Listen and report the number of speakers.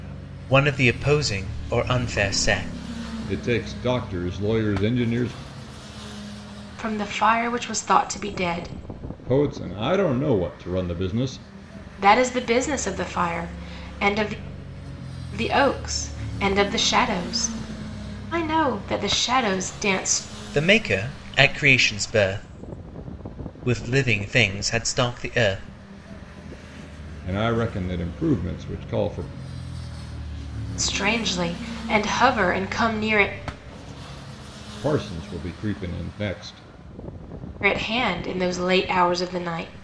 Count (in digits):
3